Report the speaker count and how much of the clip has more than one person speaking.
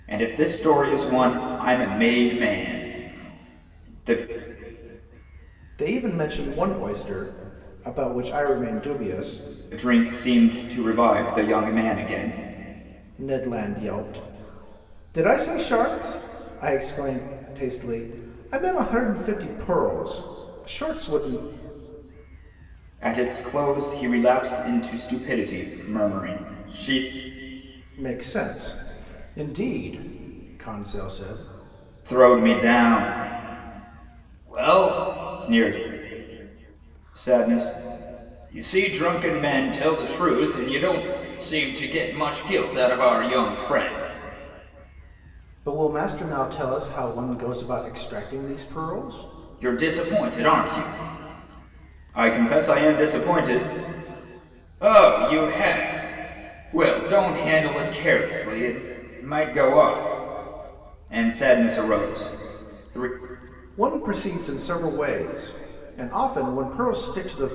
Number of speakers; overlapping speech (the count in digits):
2, no overlap